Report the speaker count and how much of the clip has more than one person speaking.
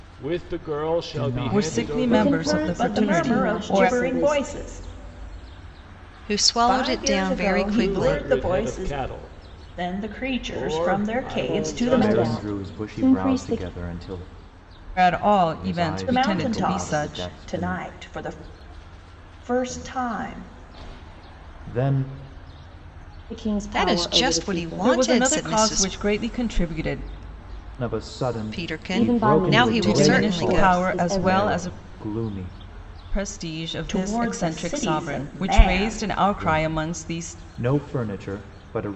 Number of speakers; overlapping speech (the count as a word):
six, about 54%